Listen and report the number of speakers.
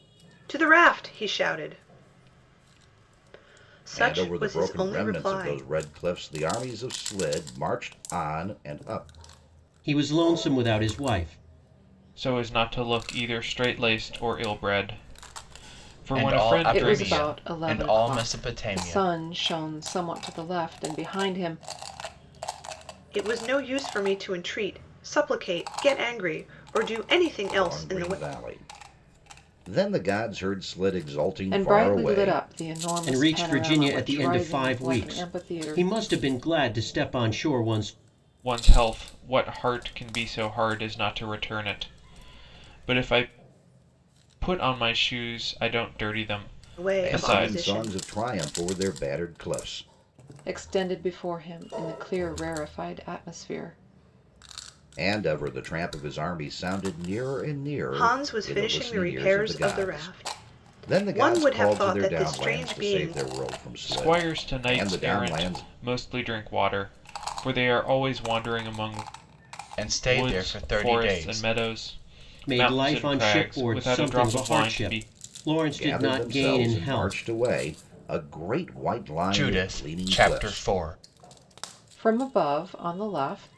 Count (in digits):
6